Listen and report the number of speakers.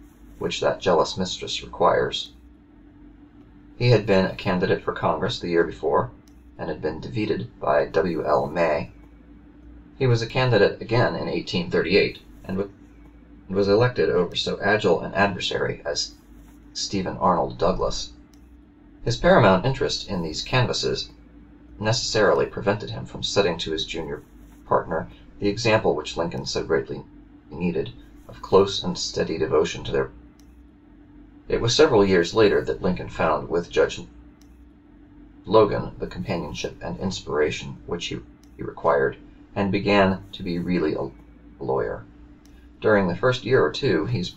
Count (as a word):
one